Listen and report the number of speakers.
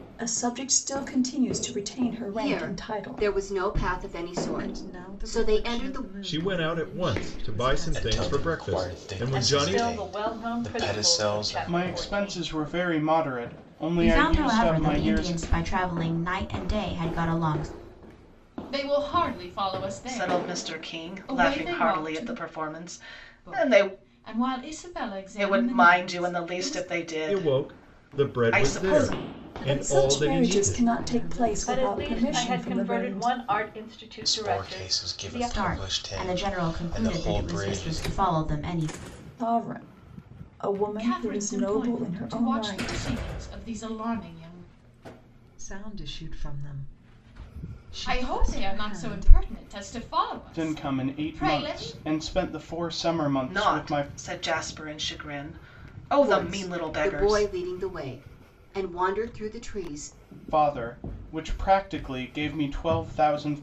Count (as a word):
ten